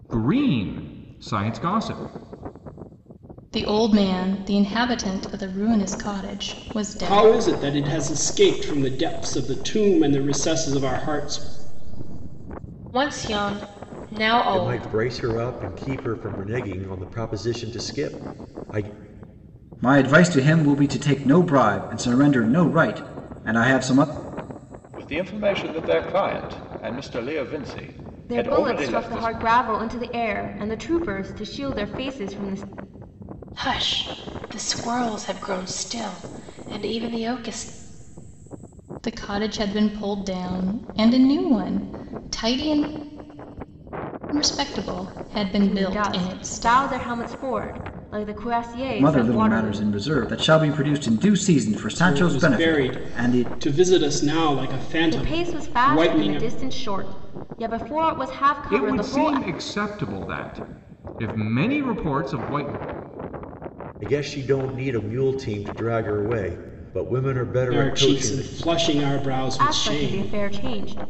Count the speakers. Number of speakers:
8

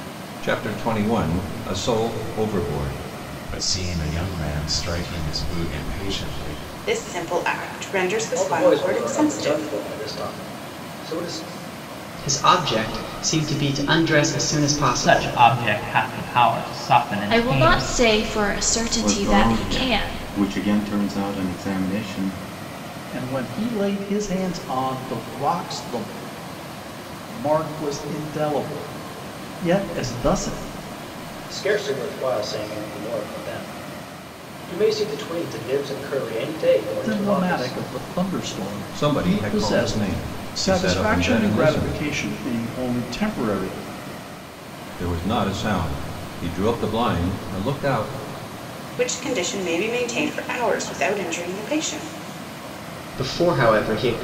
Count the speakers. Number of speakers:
9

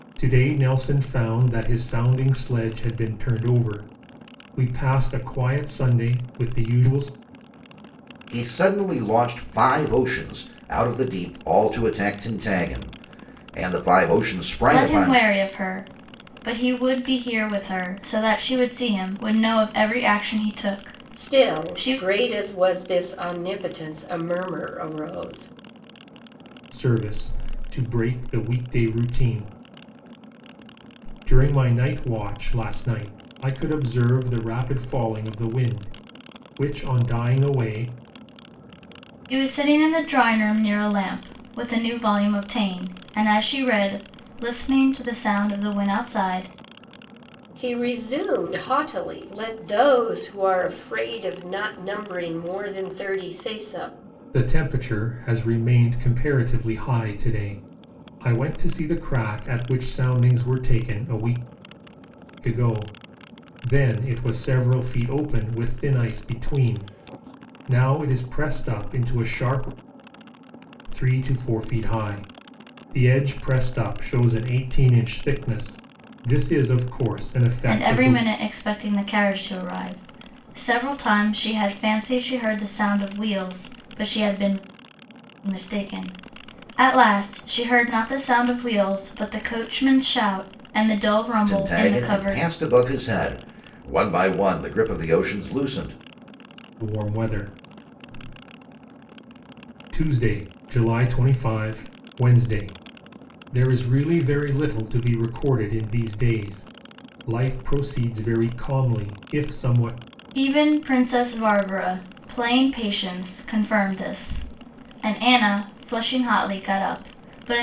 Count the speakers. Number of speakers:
4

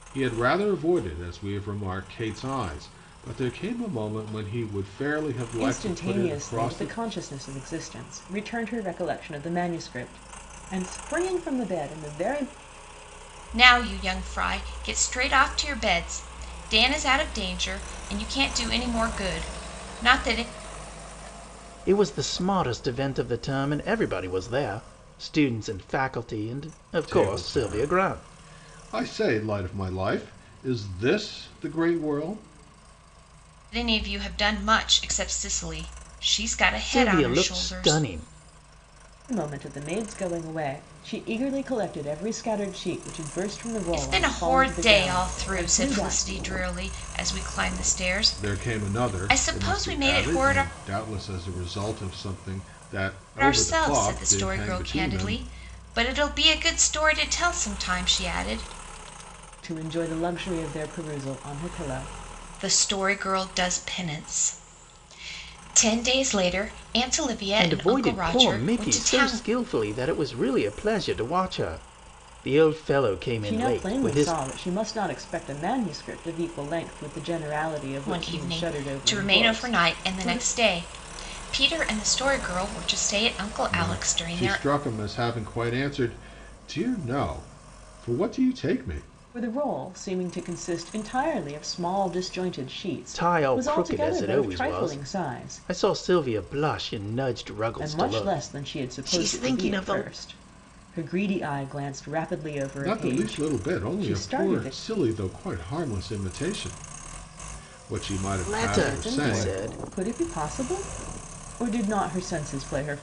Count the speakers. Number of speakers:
4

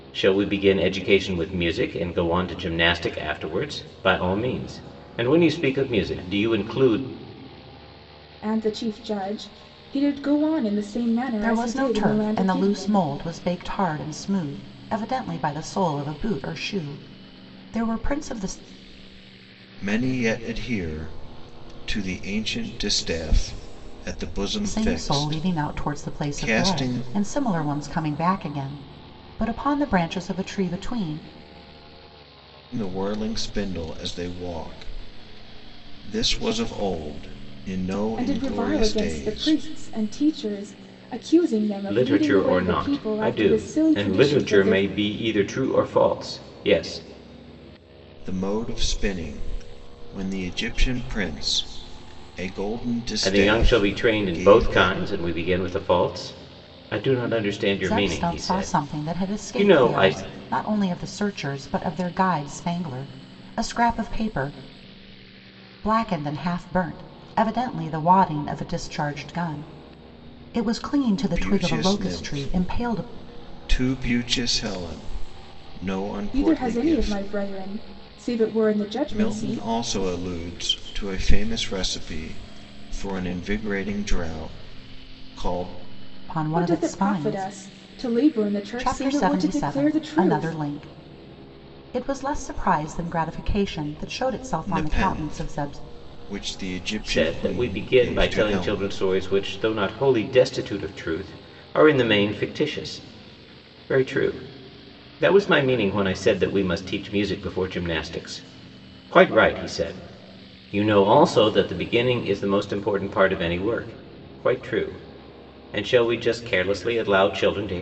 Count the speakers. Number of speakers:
4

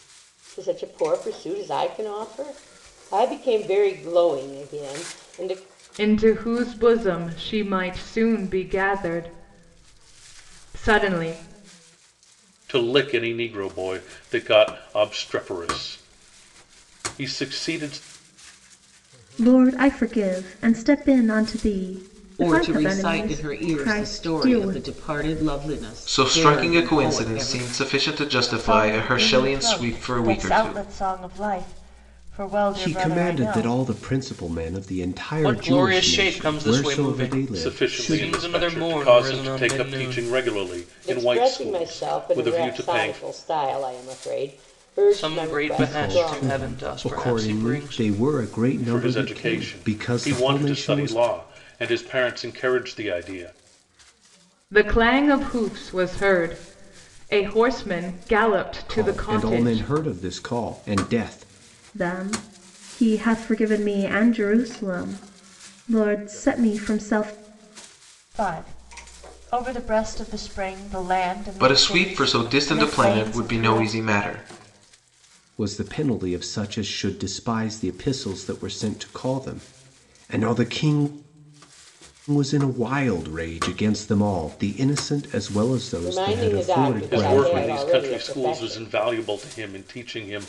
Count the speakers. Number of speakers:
9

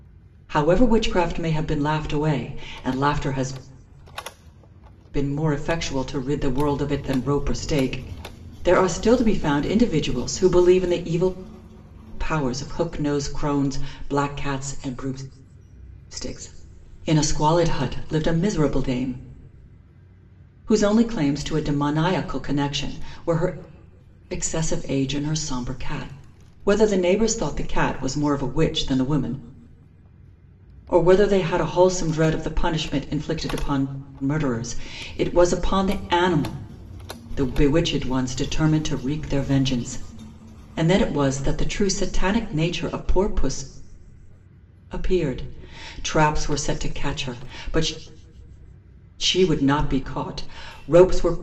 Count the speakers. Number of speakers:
1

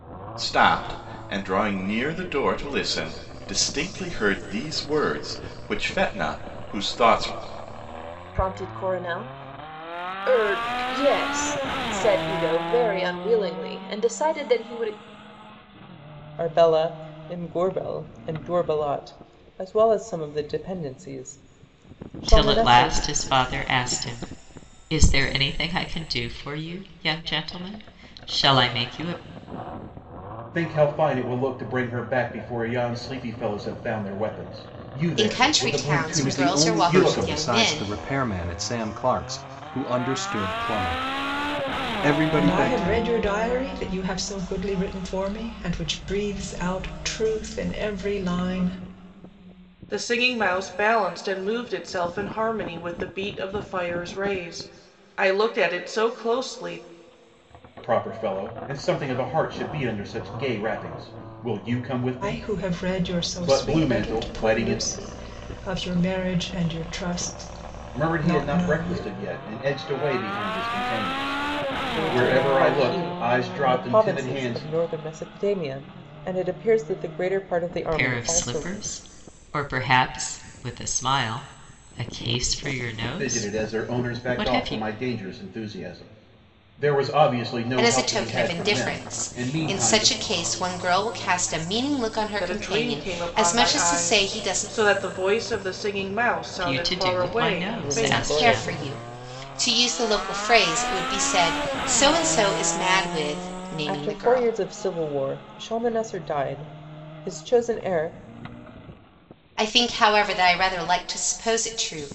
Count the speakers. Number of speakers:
9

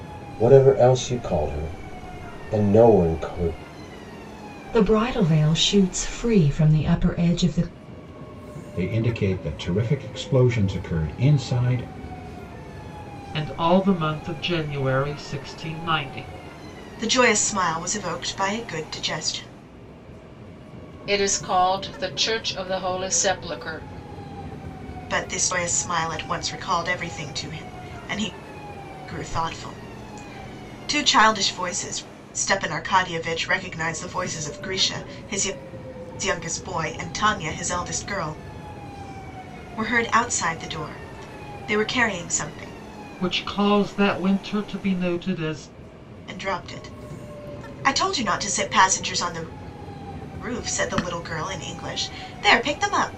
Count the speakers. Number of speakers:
6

